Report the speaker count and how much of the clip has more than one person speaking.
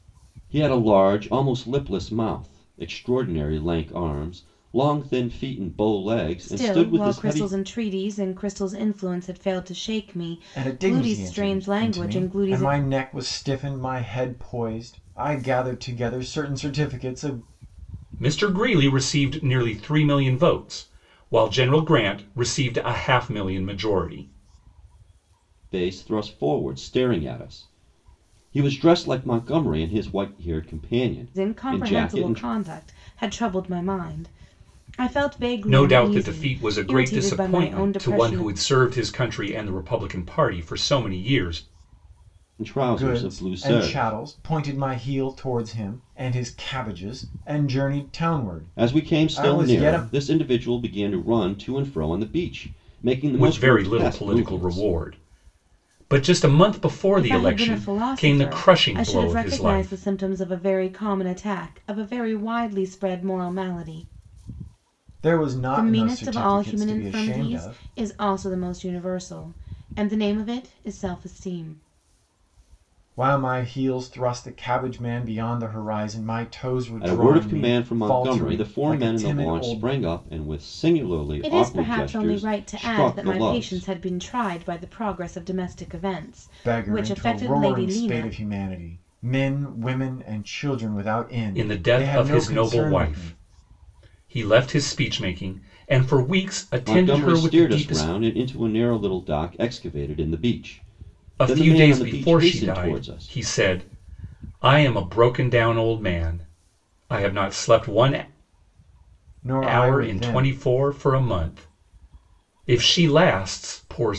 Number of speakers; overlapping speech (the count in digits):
4, about 26%